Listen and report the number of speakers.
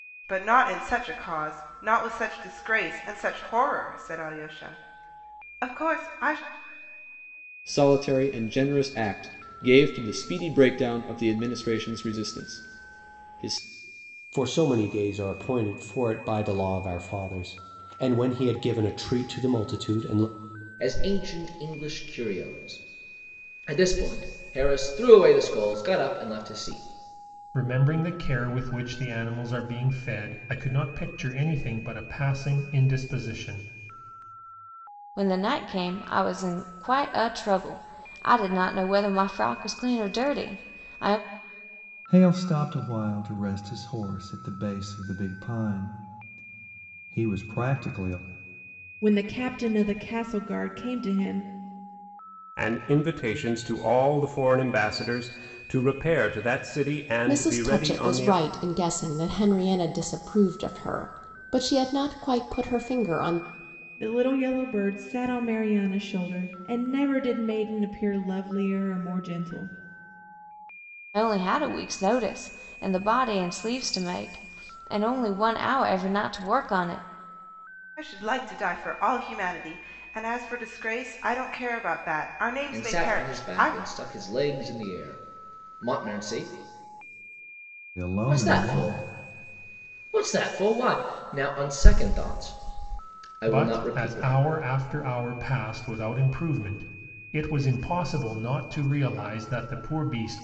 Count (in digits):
10